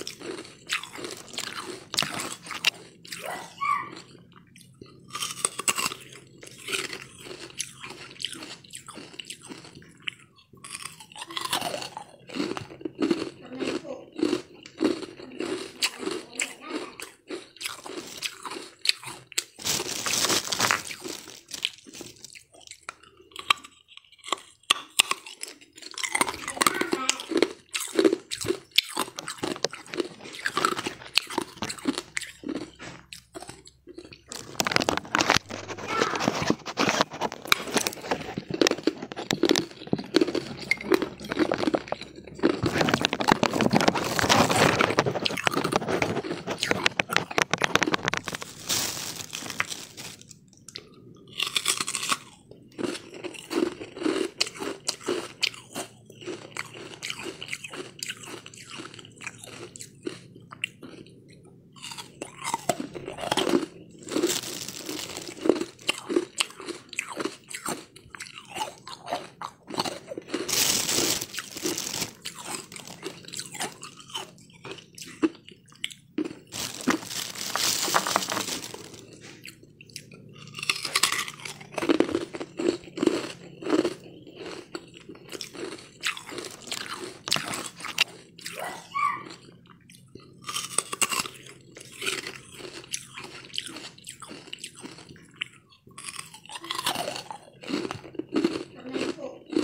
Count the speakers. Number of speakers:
0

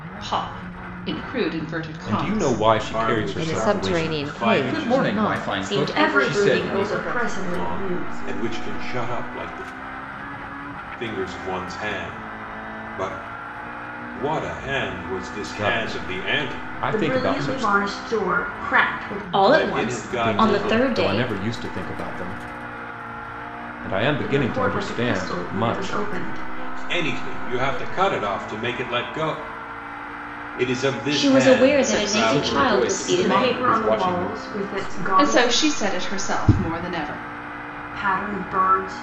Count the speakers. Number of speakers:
8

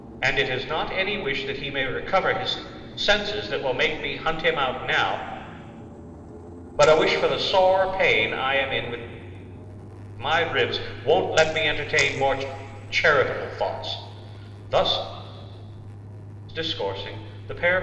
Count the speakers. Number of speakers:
1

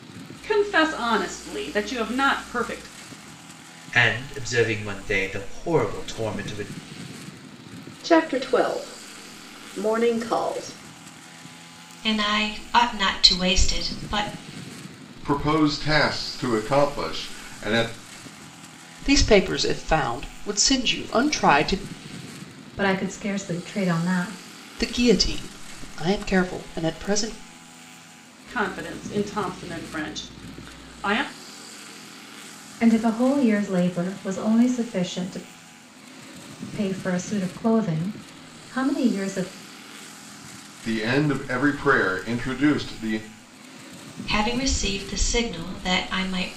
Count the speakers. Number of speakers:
7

